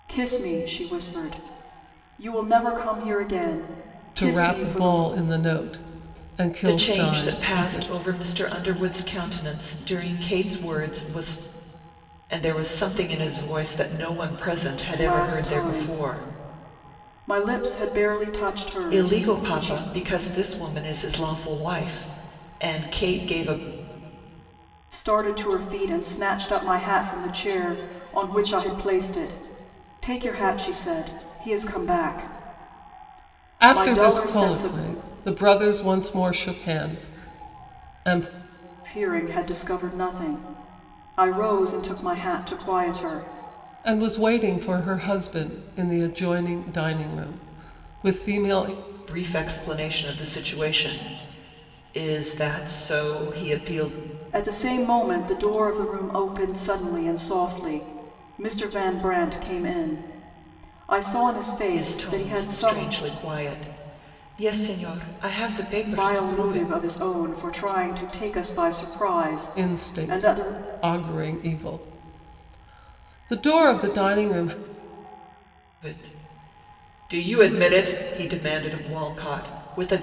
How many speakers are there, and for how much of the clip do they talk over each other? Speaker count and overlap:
three, about 11%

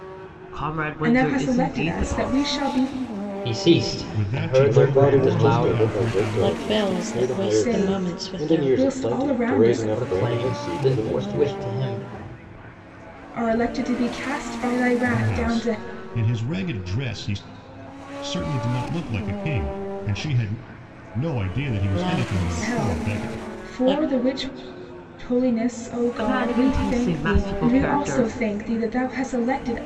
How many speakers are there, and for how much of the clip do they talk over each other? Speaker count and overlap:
six, about 47%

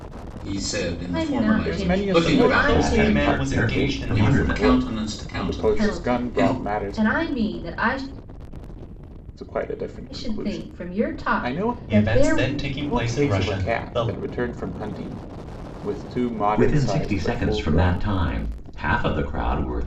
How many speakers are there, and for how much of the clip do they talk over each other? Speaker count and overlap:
five, about 55%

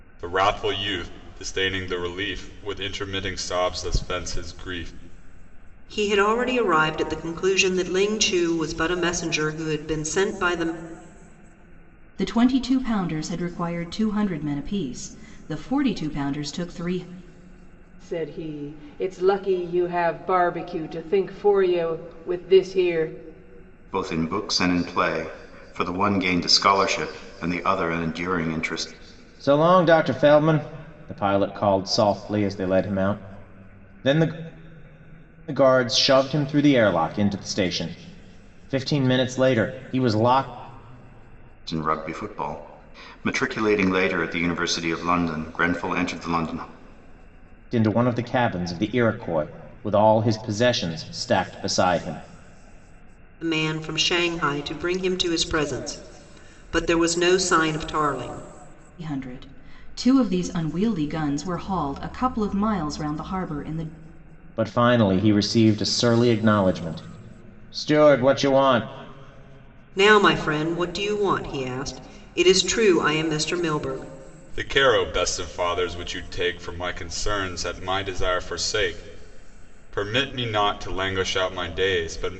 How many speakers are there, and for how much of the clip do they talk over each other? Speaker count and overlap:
six, no overlap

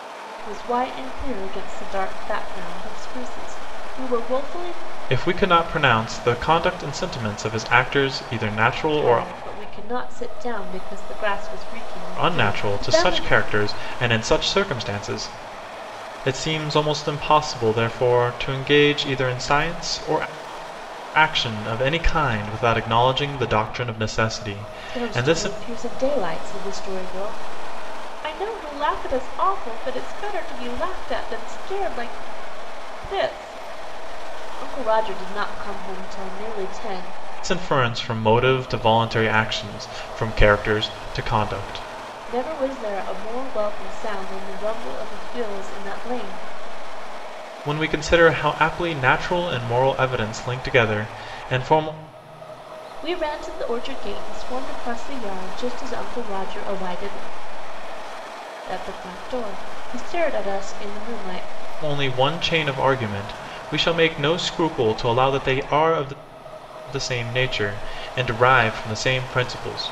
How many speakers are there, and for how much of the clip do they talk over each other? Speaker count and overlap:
two, about 3%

